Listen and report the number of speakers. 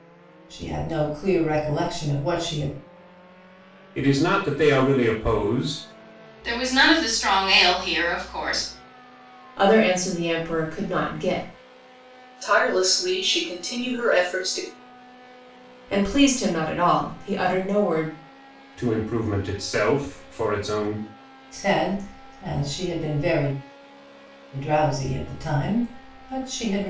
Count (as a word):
five